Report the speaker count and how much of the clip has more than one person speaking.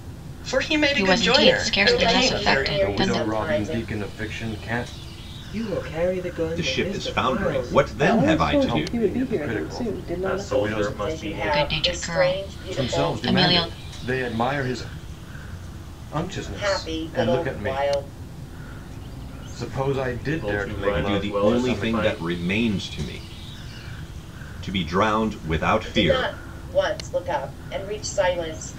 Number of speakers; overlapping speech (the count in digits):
7, about 47%